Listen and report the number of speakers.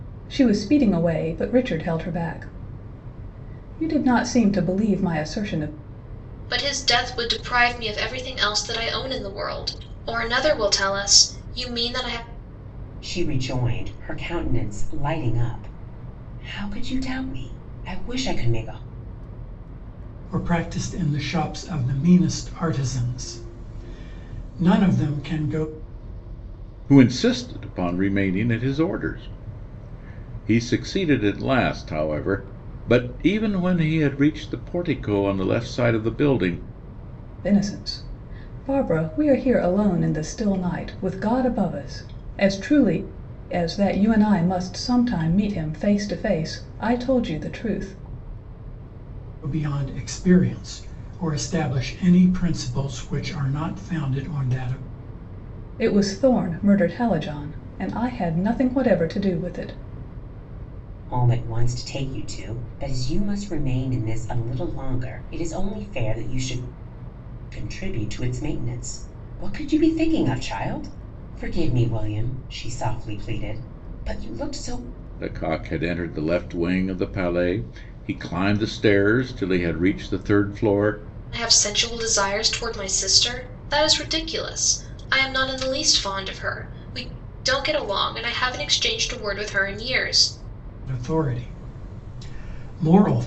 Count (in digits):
5